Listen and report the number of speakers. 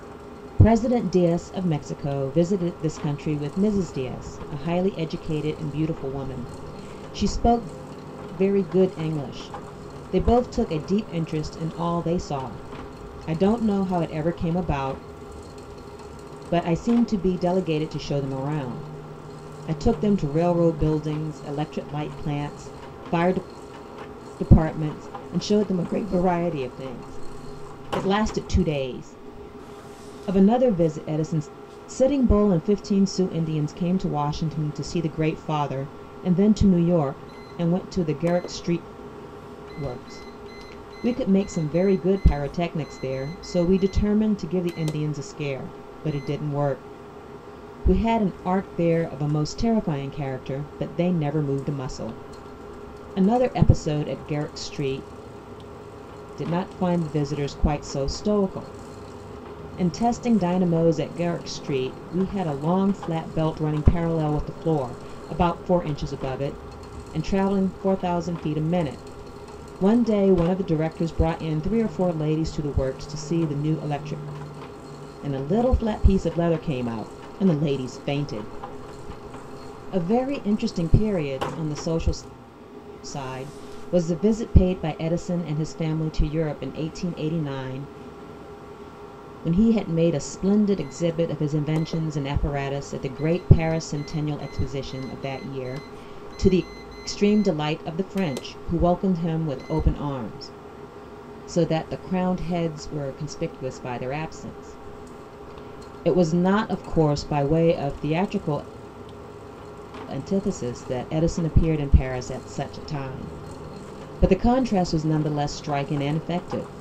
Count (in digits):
1